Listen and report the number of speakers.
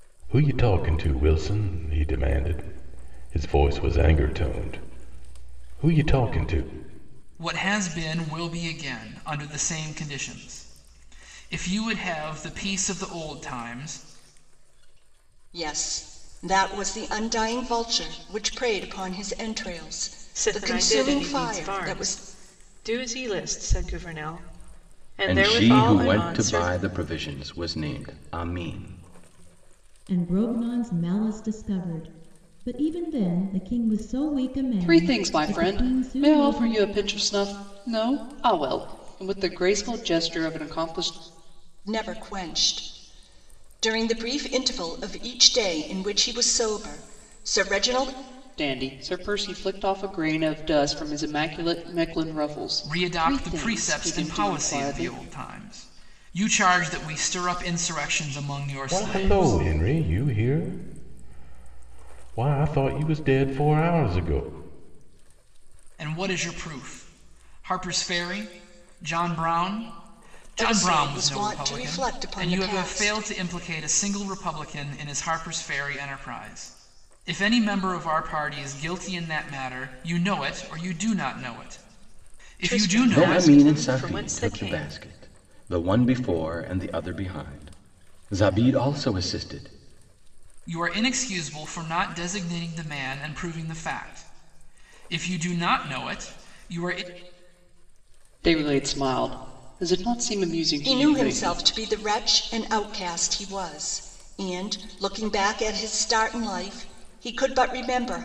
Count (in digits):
7